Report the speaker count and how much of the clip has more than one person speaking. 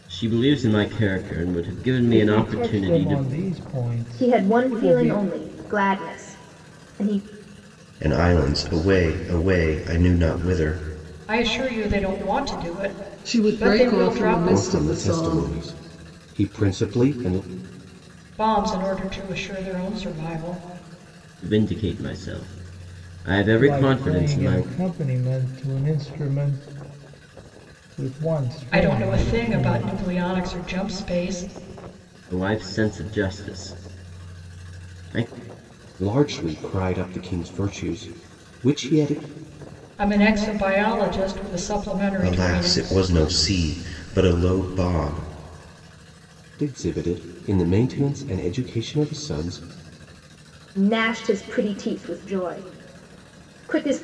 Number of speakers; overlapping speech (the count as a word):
seven, about 14%